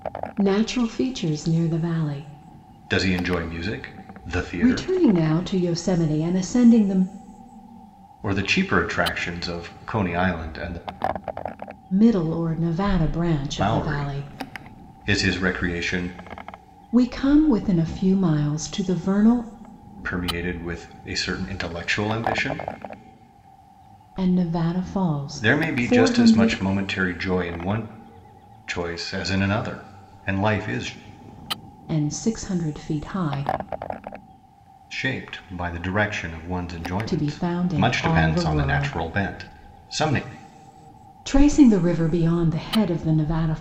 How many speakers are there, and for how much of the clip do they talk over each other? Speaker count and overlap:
2, about 9%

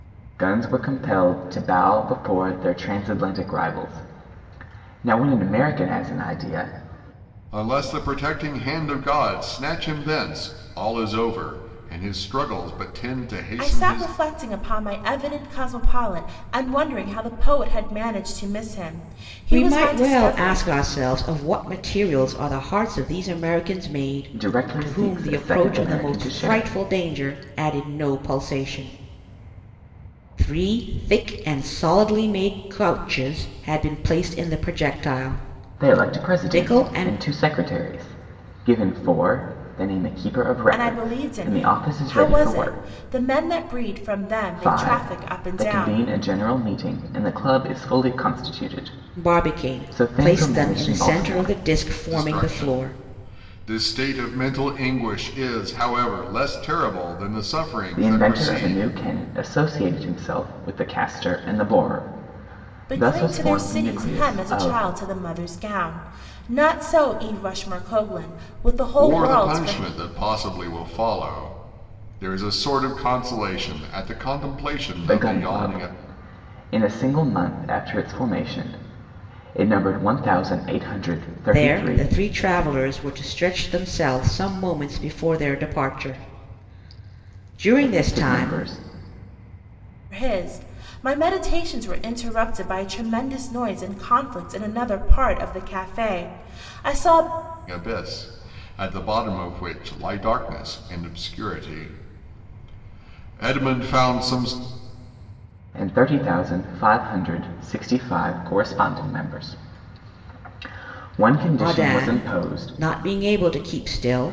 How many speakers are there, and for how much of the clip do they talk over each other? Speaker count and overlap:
4, about 18%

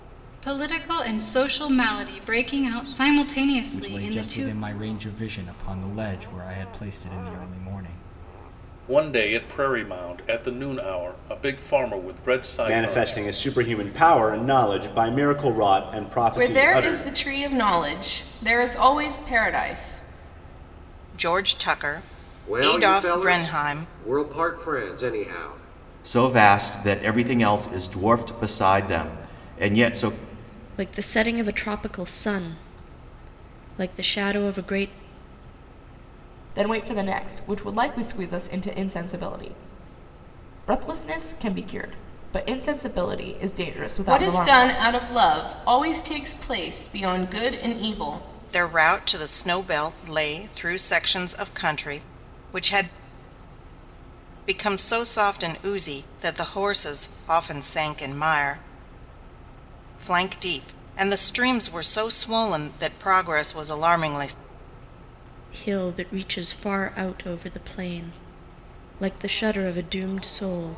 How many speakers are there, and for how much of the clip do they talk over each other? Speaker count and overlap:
10, about 7%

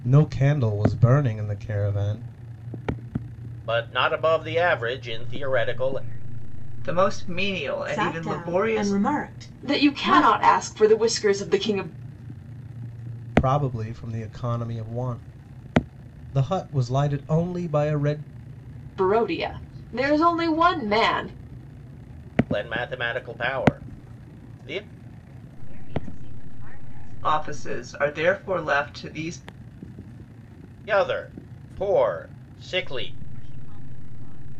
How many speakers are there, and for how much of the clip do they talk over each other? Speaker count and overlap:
6, about 13%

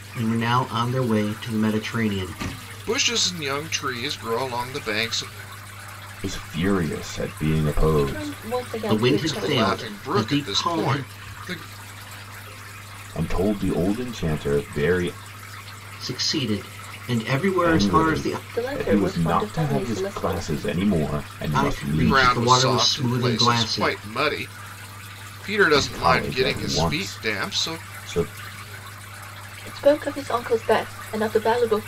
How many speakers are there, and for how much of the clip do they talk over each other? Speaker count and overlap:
4, about 31%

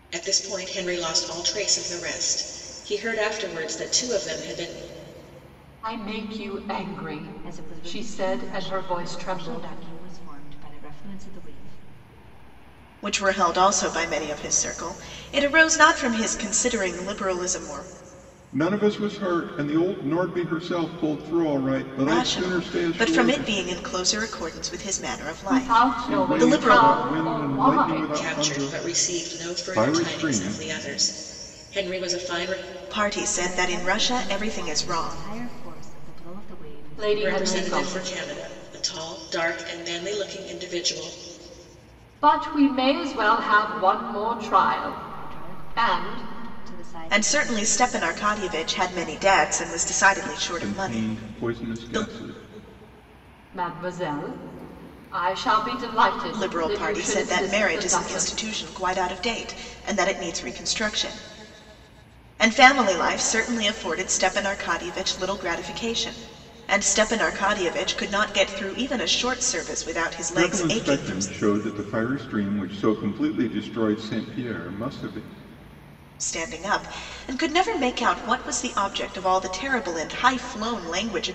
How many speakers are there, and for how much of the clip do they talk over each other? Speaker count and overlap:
5, about 23%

